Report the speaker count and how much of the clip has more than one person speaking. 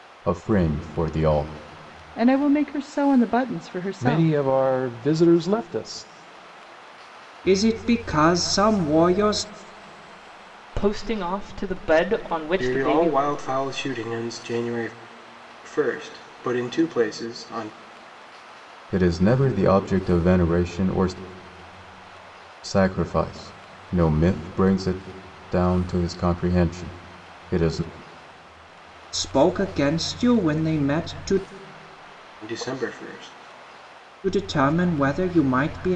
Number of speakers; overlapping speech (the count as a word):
six, about 3%